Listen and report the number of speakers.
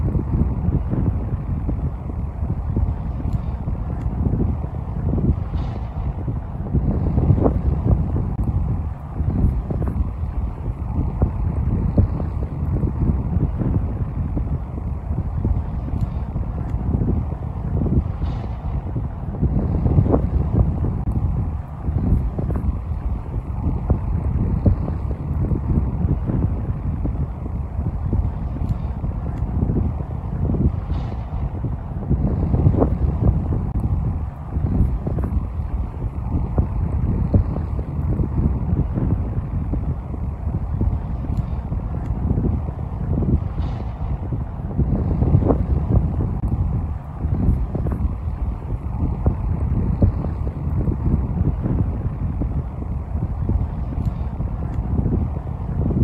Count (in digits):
0